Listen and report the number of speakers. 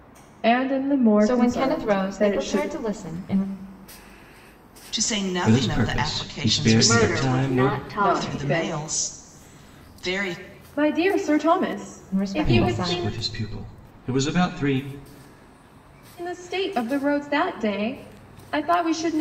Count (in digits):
5